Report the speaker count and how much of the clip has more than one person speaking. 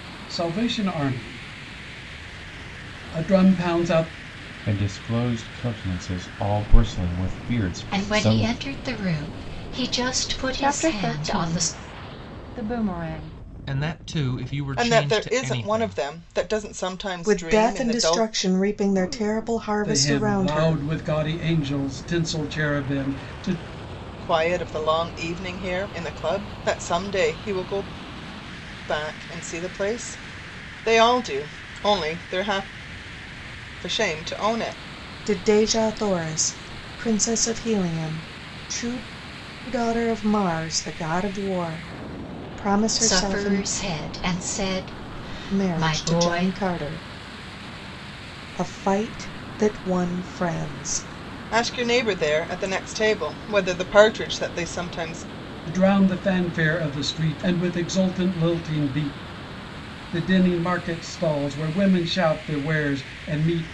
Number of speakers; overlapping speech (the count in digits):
7, about 11%